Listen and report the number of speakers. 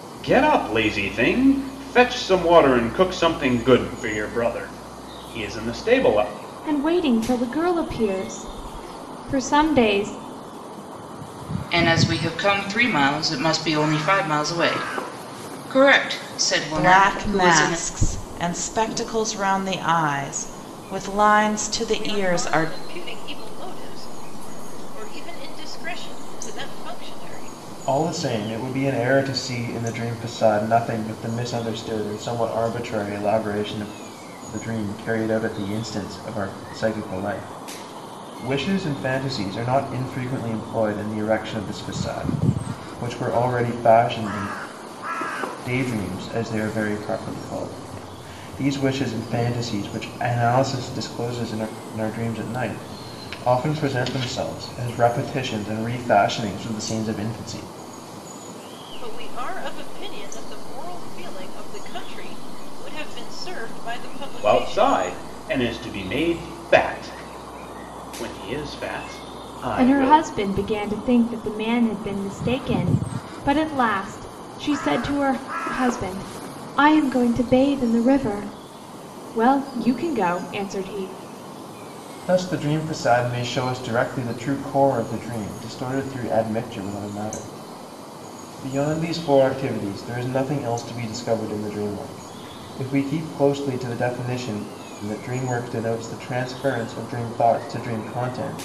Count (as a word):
six